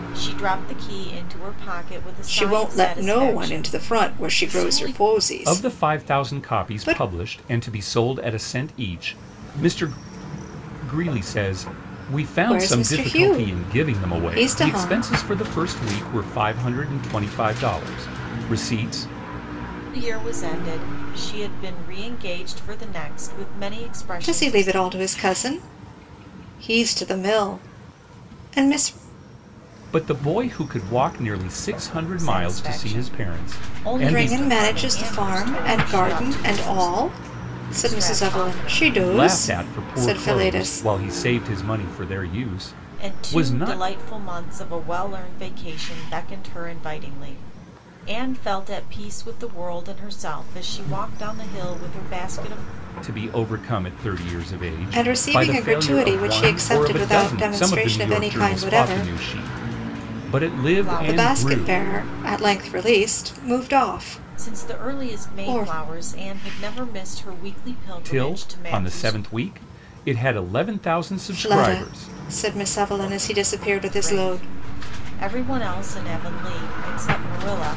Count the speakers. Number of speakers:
three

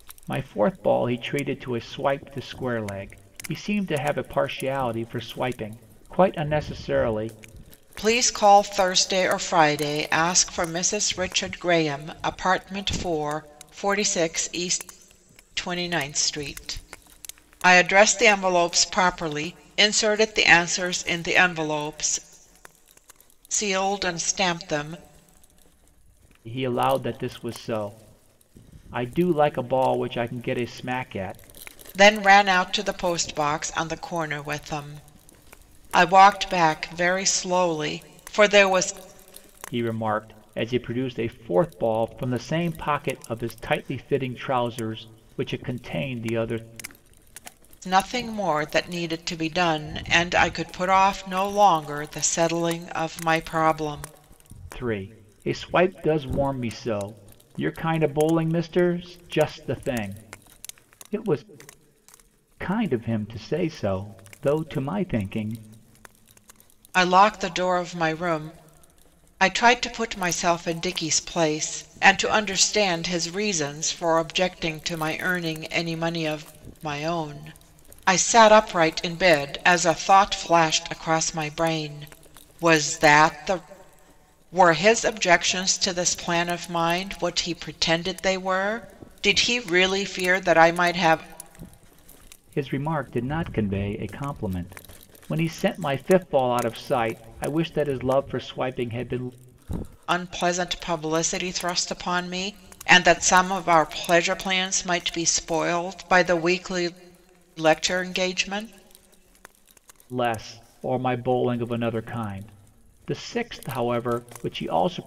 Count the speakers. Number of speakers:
two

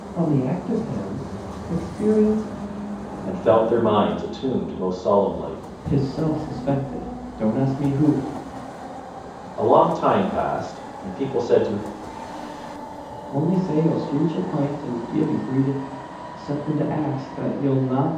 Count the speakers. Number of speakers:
three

